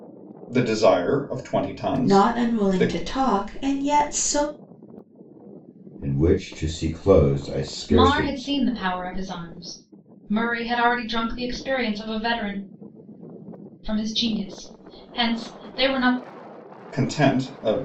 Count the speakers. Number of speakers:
four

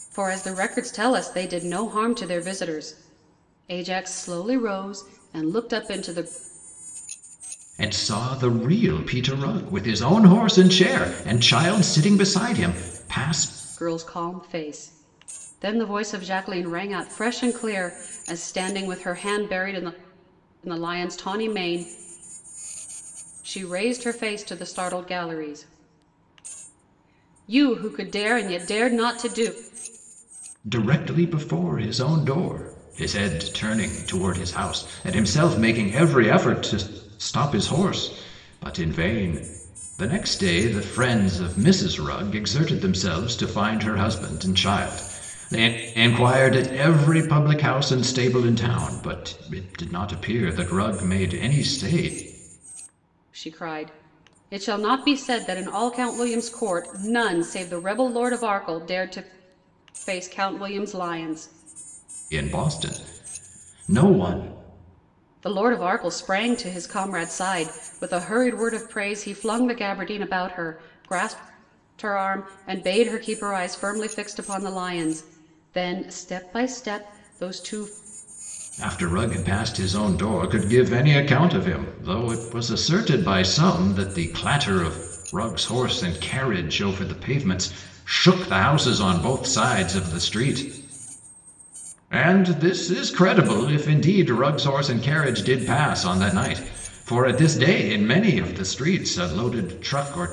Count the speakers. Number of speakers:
two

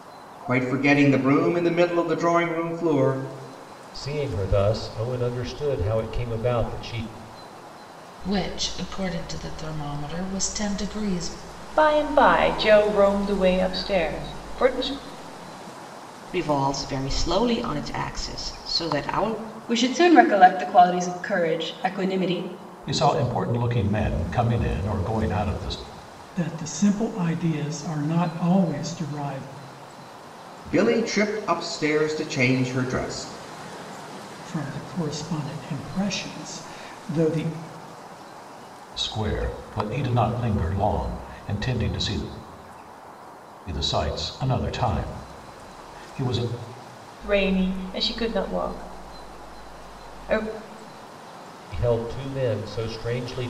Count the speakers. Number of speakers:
eight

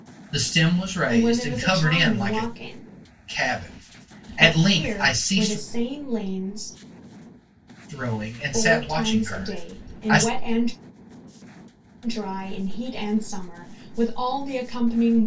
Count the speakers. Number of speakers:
two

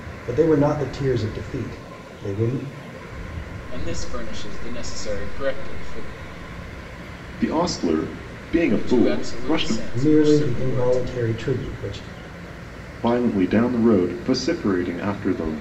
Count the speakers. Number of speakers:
three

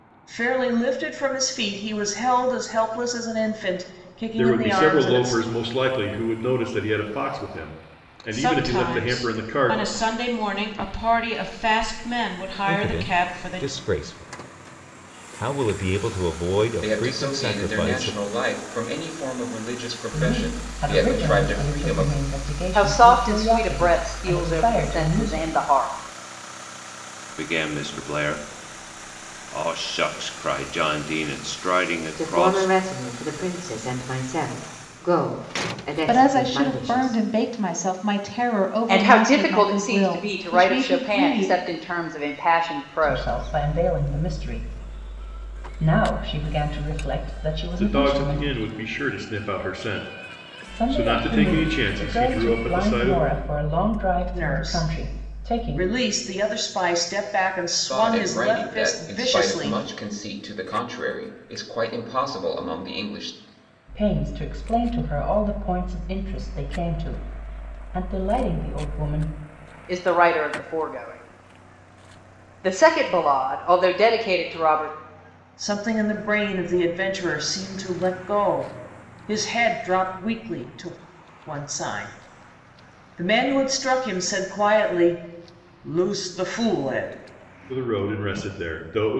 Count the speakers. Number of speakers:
ten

